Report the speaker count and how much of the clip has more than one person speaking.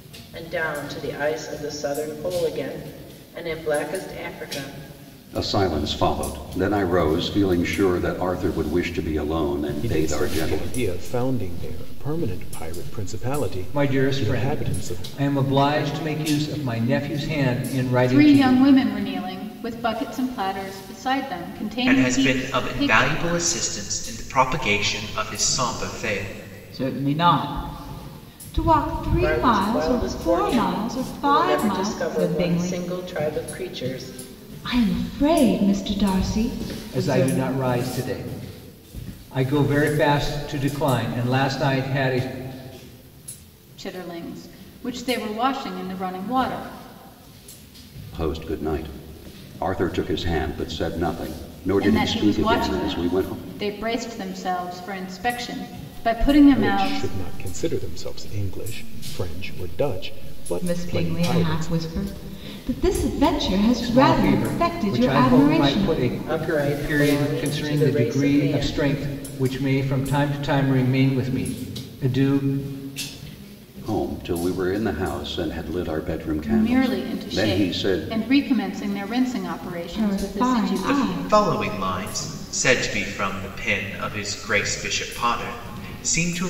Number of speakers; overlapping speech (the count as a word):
seven, about 25%